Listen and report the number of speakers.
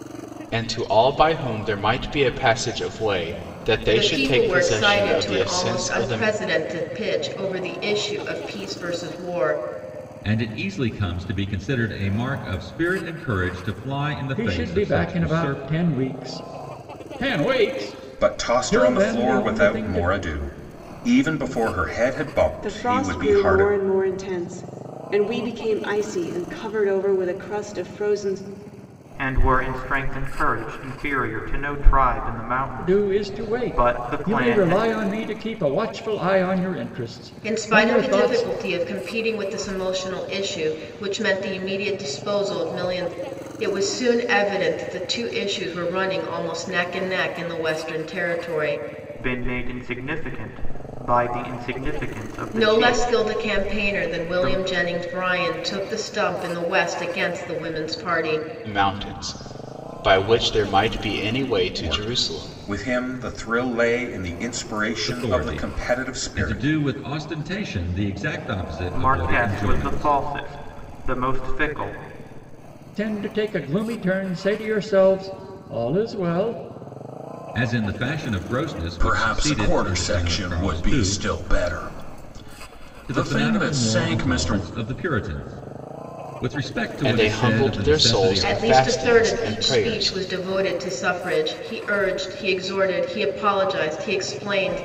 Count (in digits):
7